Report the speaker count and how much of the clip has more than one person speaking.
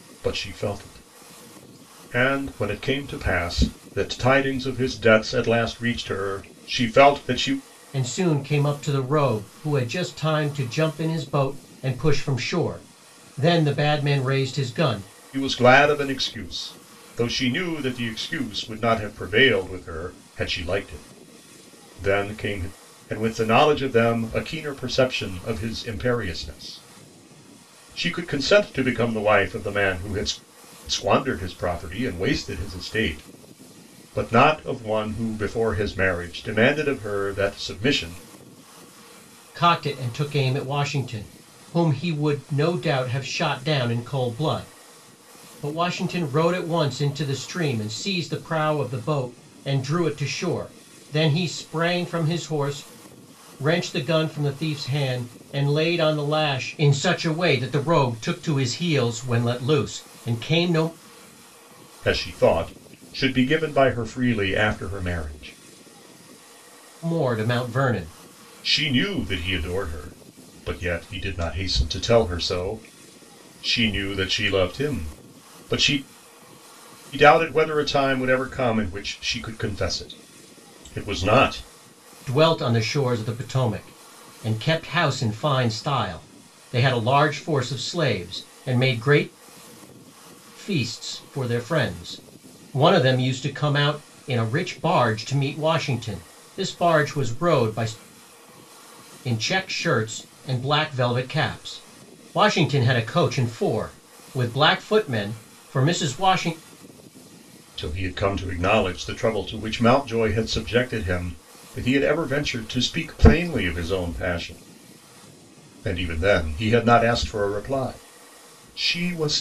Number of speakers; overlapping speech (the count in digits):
2, no overlap